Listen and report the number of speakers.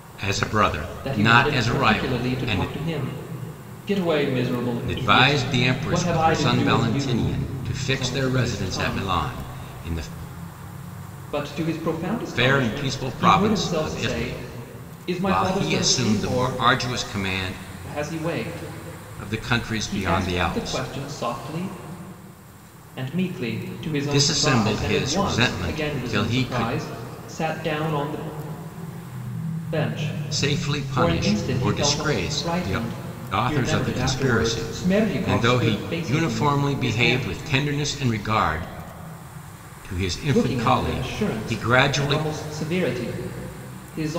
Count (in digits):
2